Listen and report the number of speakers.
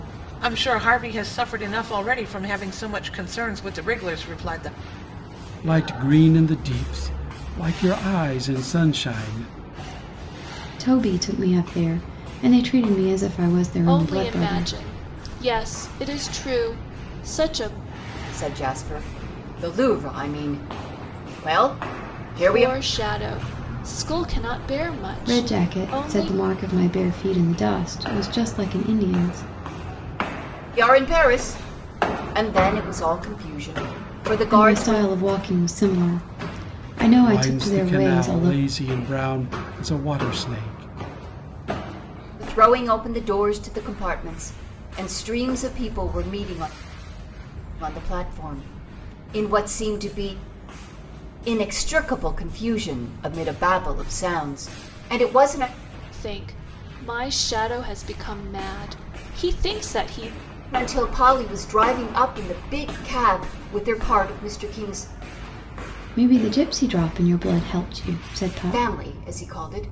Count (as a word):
five